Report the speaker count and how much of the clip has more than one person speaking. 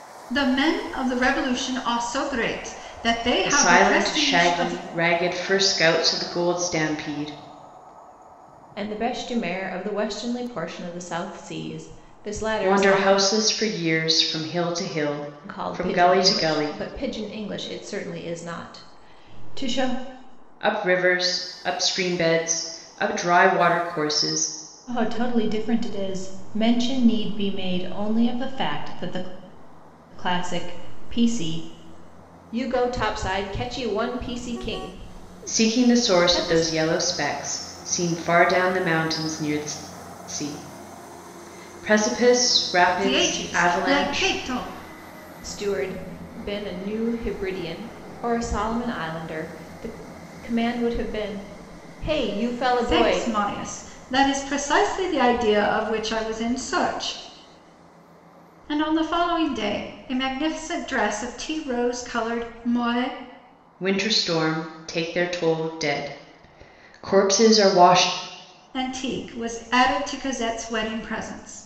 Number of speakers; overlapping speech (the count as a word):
three, about 9%